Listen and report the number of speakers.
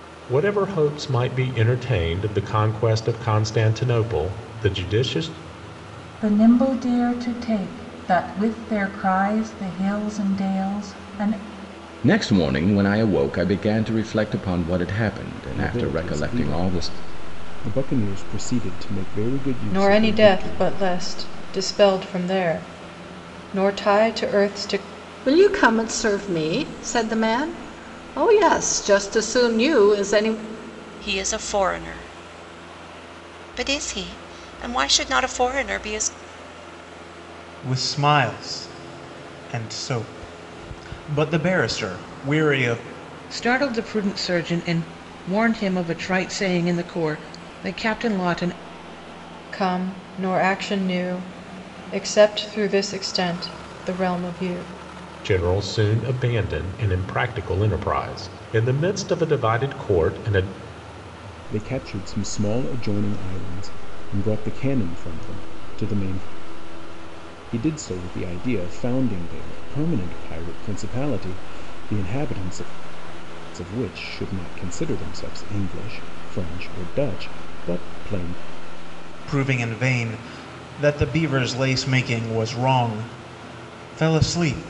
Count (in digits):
9